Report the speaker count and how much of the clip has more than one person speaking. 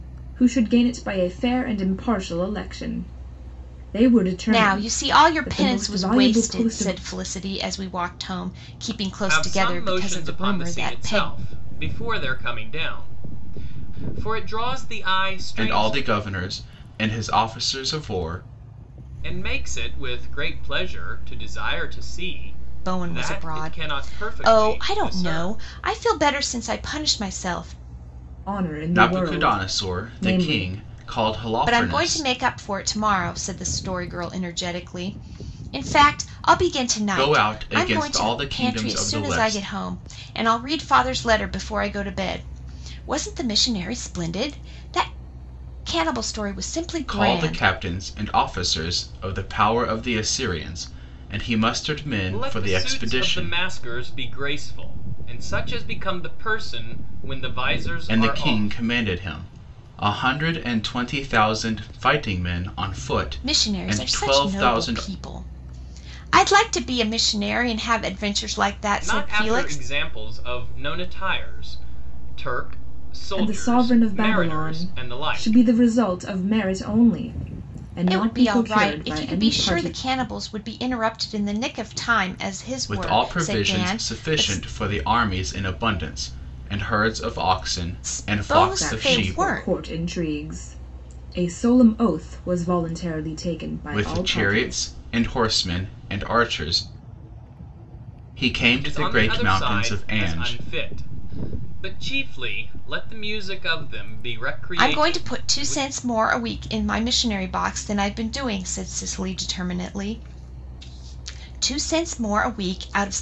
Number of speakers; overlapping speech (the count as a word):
four, about 27%